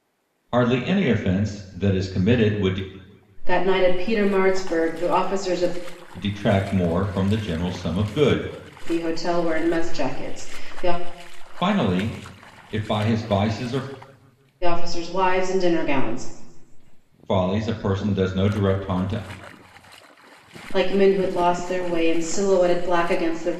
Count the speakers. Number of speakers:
two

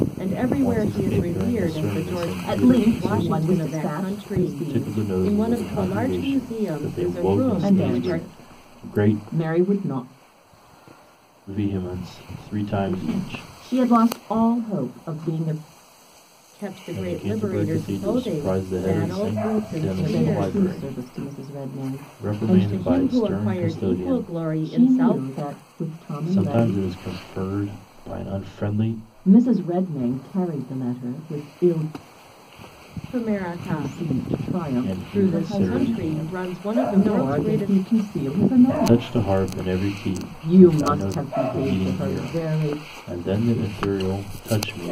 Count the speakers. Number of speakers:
three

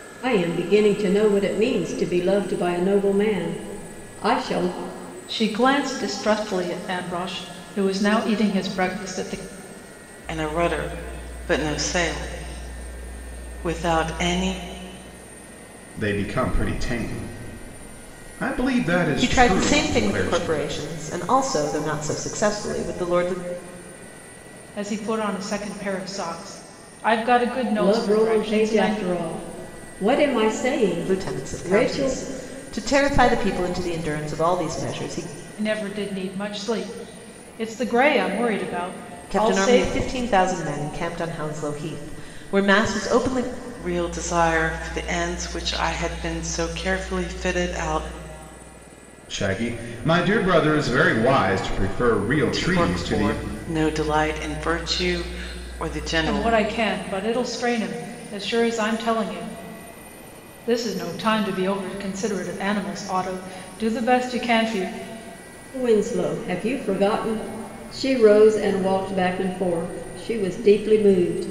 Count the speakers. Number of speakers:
five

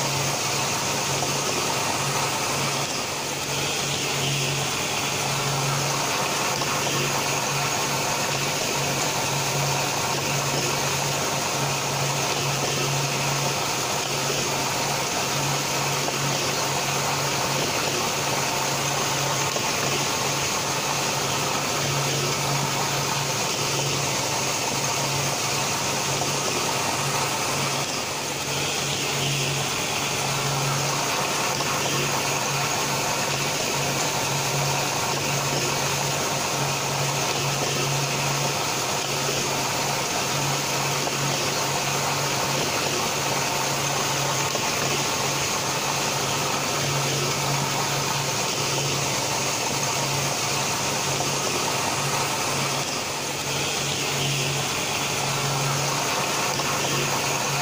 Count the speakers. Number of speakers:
zero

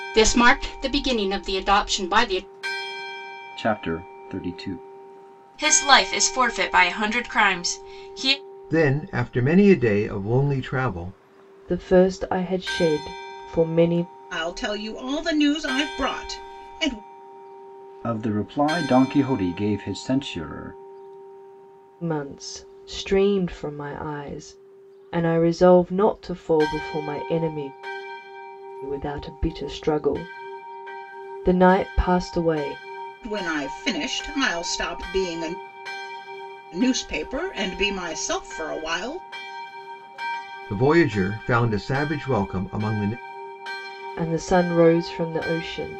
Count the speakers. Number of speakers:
six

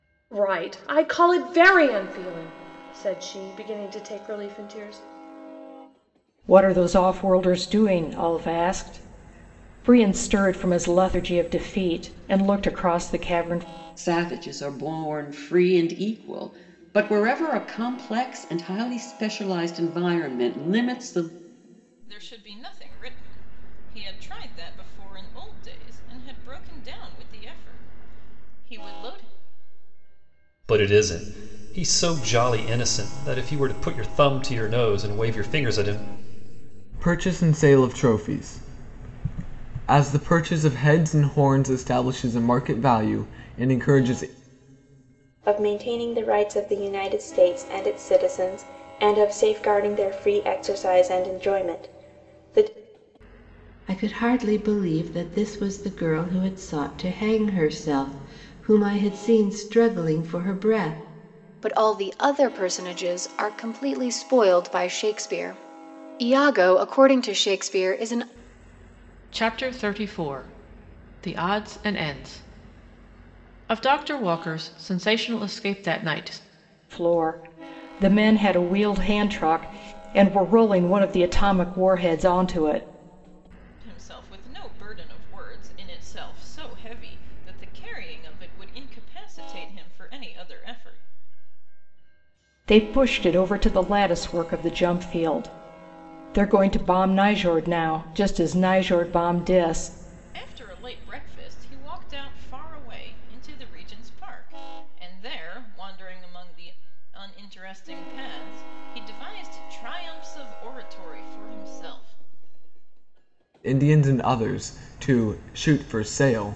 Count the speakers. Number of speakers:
ten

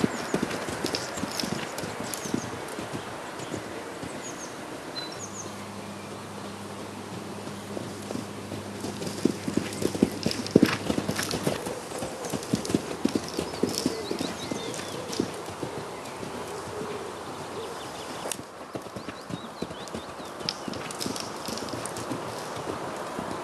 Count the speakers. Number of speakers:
zero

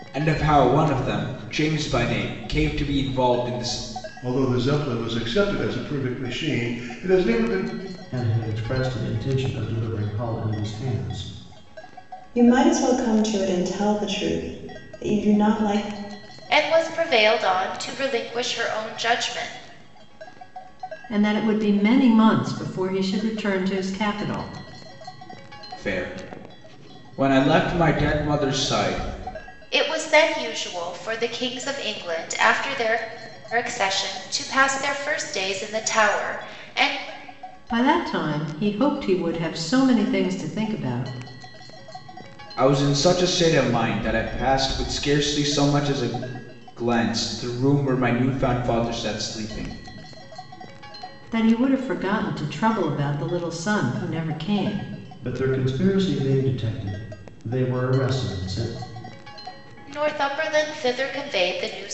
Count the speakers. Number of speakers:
six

